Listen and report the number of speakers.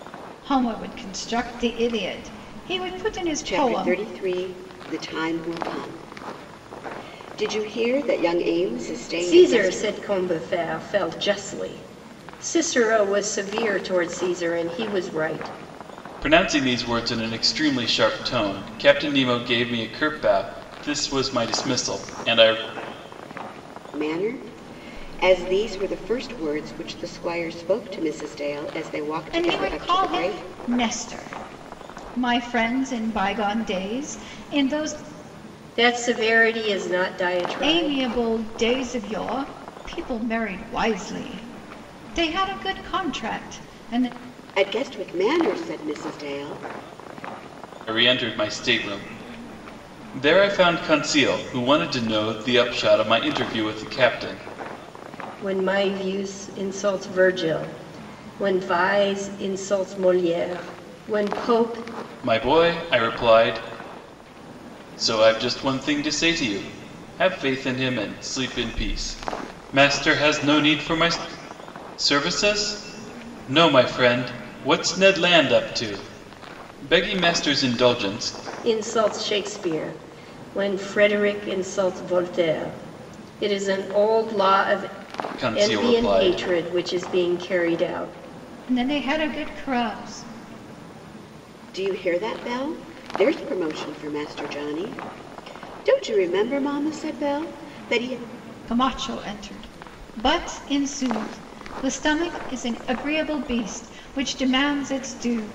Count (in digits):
4